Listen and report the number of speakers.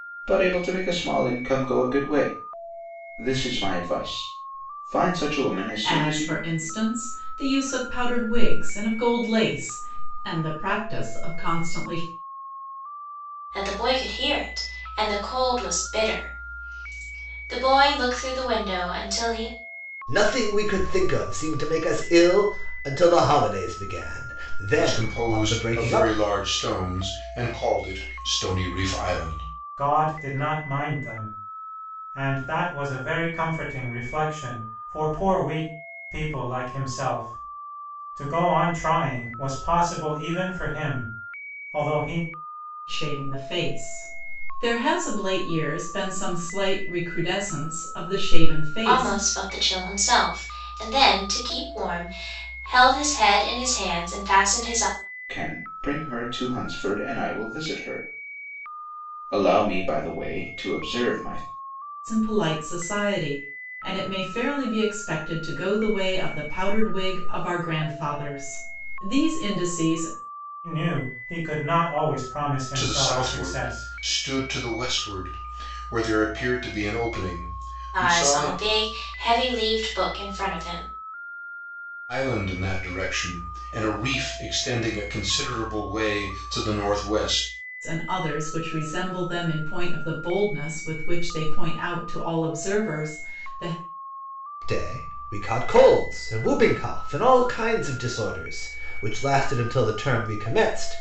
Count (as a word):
six